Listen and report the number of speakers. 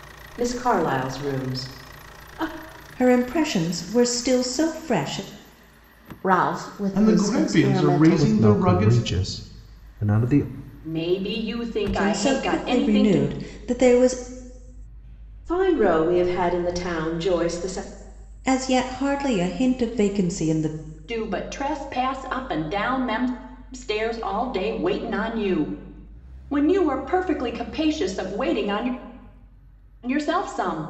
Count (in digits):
6